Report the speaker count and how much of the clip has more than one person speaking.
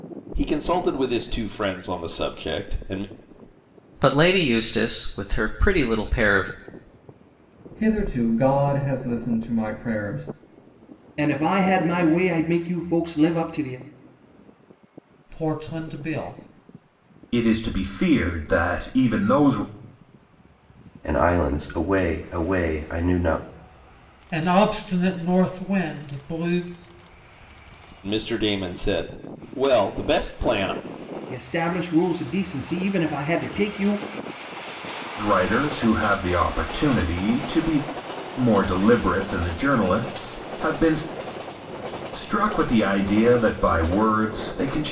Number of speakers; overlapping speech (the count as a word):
seven, no overlap